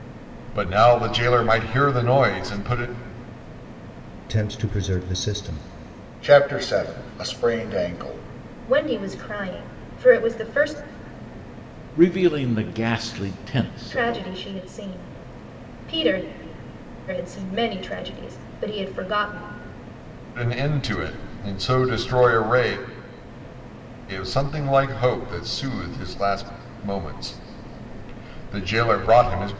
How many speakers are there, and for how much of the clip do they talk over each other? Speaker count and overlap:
five, about 1%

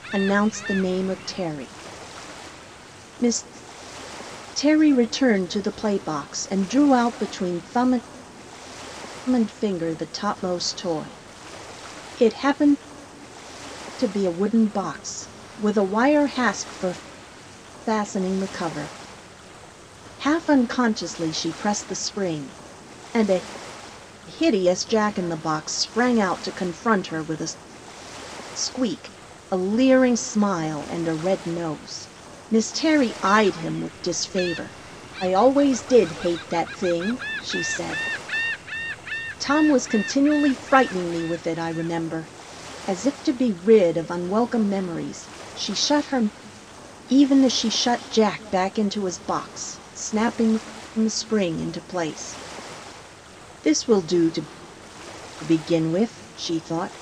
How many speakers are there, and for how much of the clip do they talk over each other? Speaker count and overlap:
one, no overlap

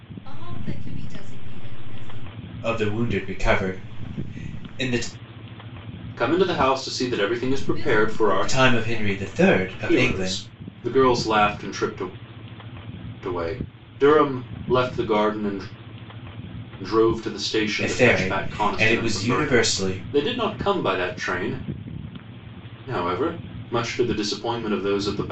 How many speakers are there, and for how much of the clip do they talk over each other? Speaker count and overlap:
three, about 18%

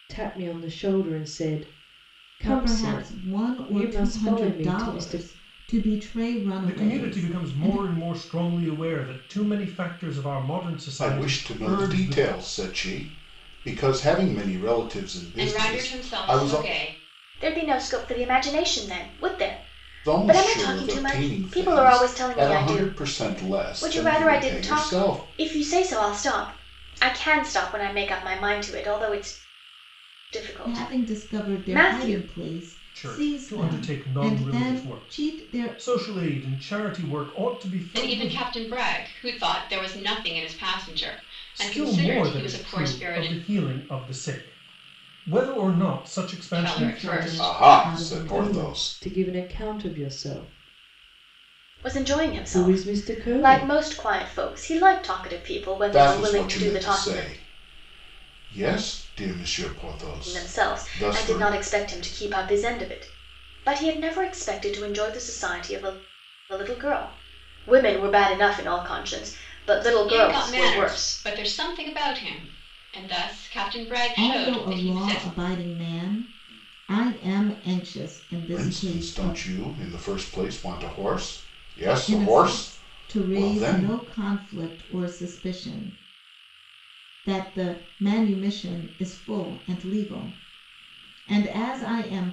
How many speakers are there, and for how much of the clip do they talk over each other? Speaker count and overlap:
six, about 33%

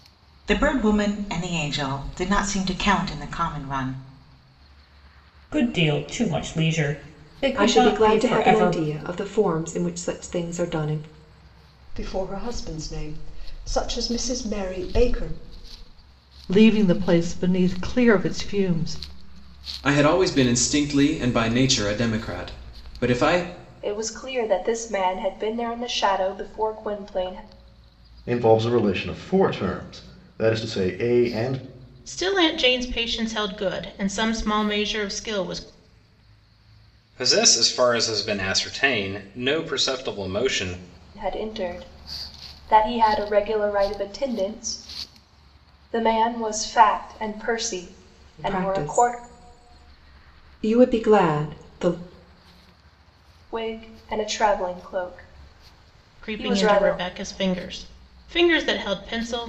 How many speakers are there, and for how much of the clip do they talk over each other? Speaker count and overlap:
ten, about 5%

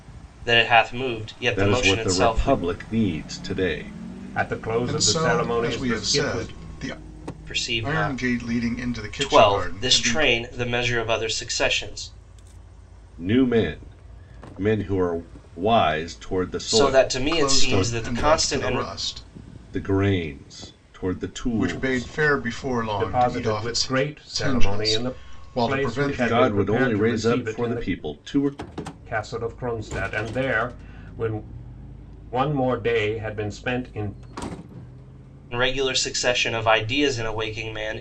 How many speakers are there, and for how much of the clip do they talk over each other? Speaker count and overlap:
four, about 32%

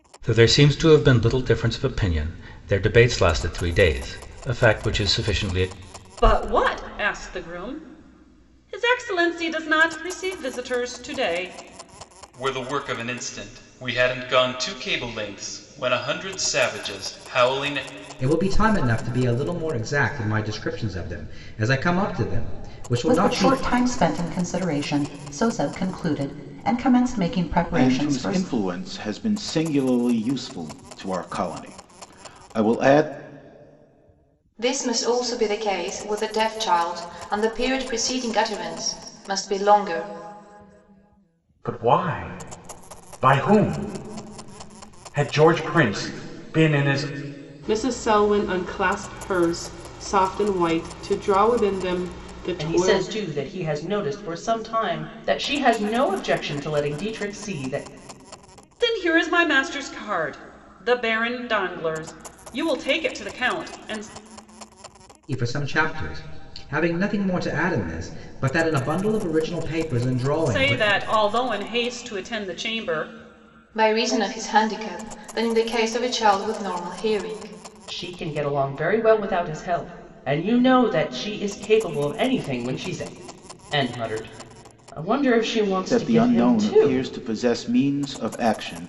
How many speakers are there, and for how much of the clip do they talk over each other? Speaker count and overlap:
ten, about 4%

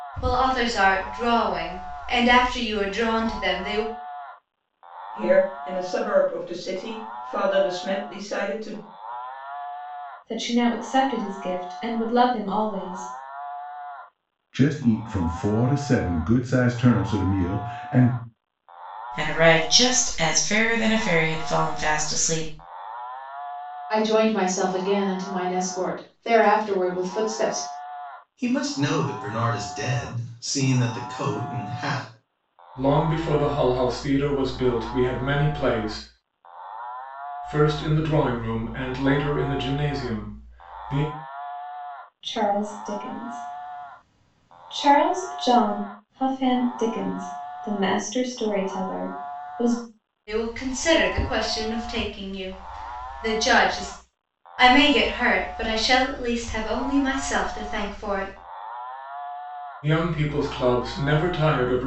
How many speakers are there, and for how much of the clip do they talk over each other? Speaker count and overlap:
eight, no overlap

